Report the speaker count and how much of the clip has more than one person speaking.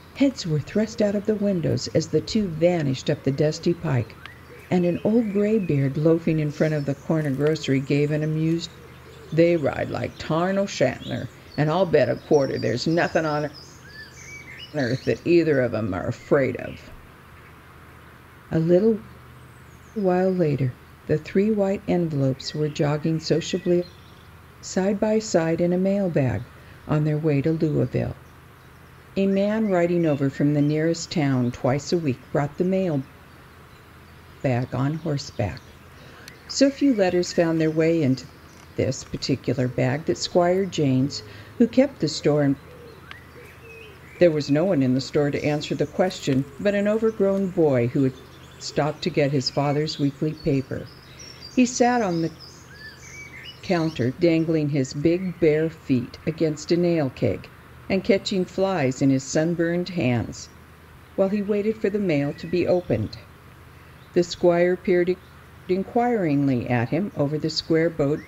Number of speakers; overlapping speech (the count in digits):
1, no overlap